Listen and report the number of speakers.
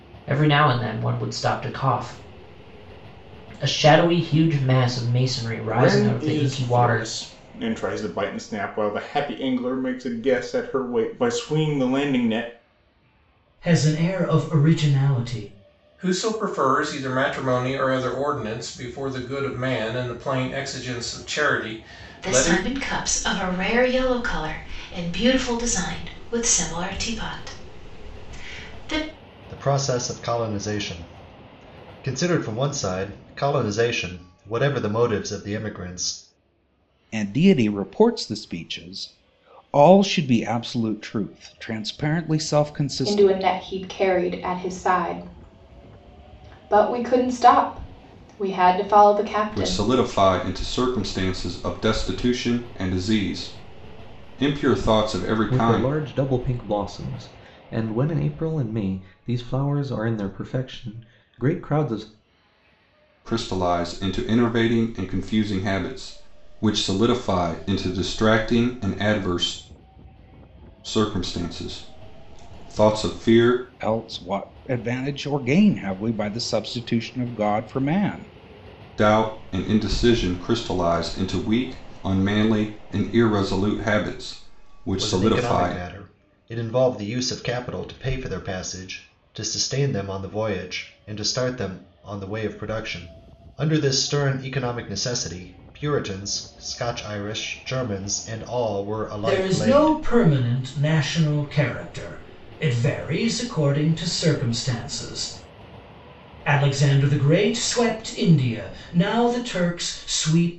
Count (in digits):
10